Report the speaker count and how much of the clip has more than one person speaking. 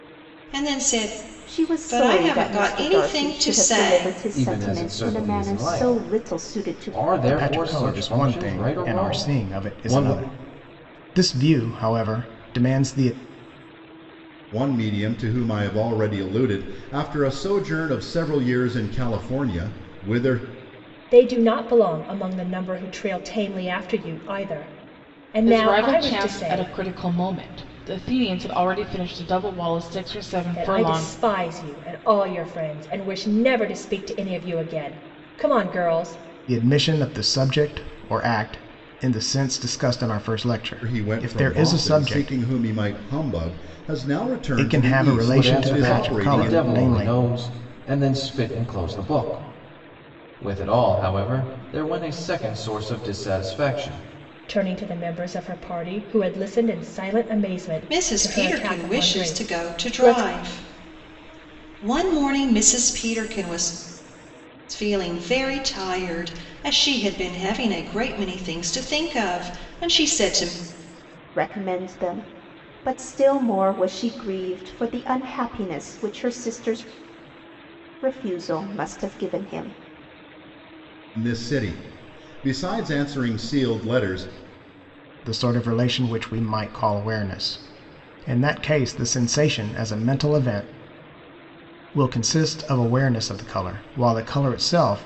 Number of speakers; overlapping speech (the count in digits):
7, about 18%